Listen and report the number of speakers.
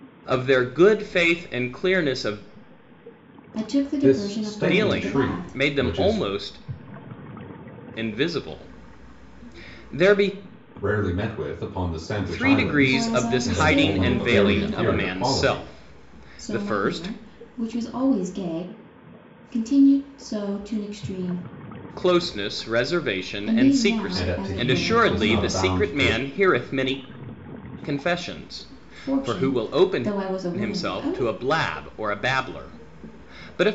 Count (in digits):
3